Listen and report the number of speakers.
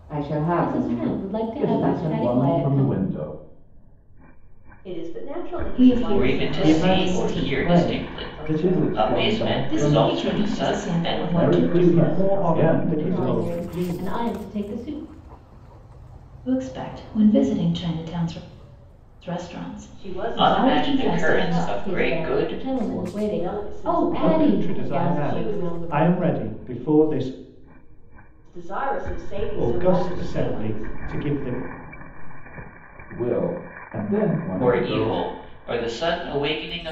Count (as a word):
seven